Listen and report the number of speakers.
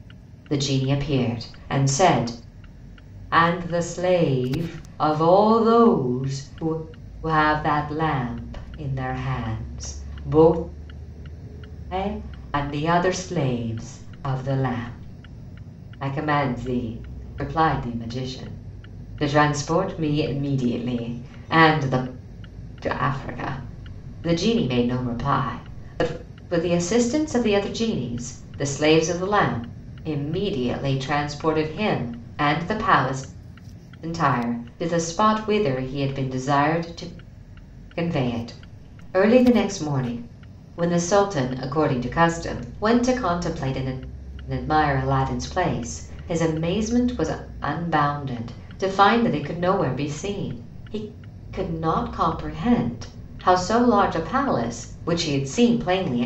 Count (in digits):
1